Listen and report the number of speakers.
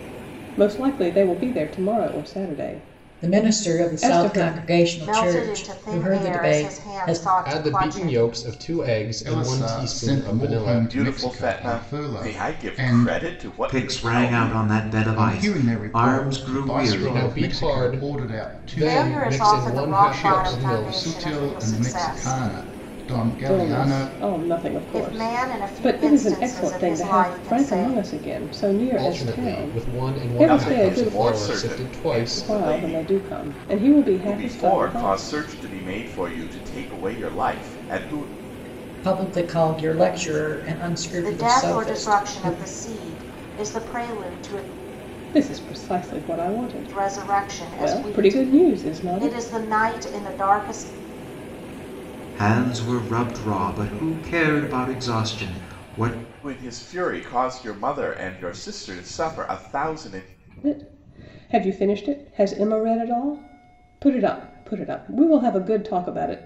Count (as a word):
seven